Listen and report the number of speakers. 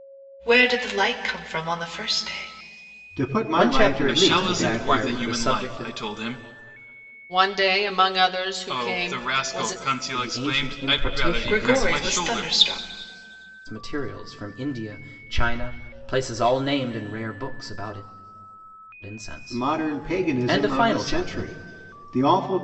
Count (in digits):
5